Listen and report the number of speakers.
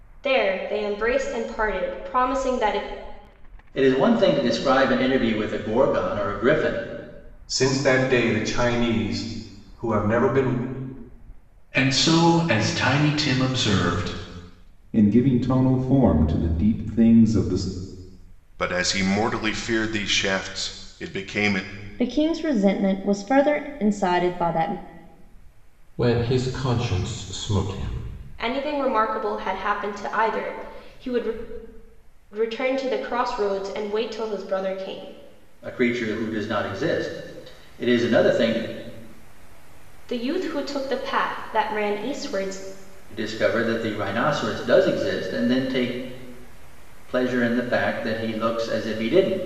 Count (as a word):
eight